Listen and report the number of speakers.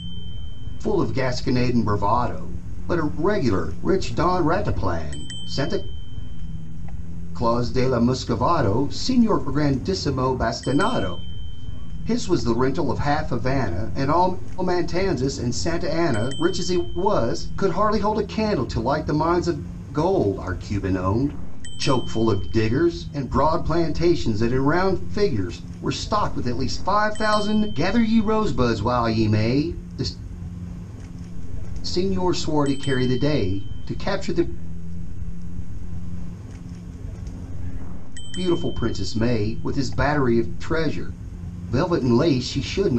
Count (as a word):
two